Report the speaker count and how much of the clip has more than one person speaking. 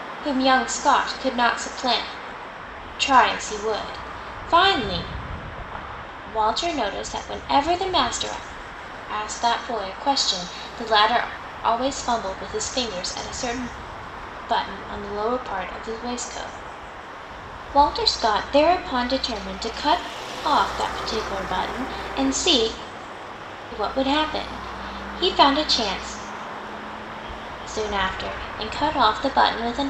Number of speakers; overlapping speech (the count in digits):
1, no overlap